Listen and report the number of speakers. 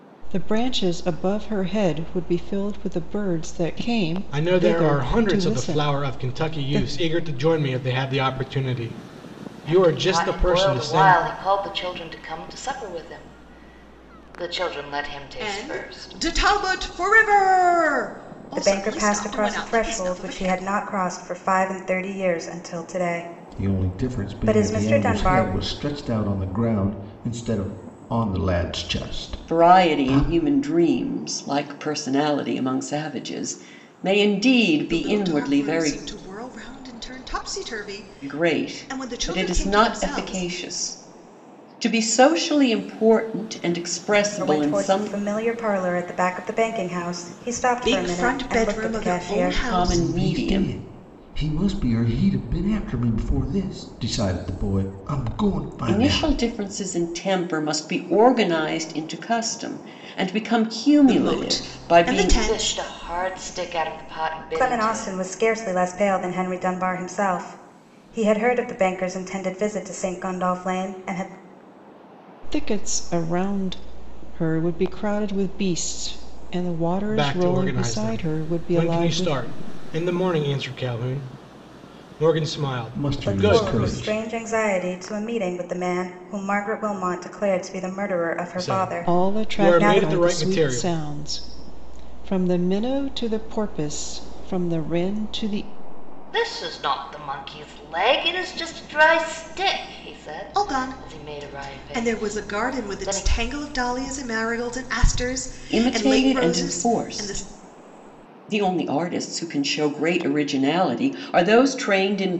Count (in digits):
7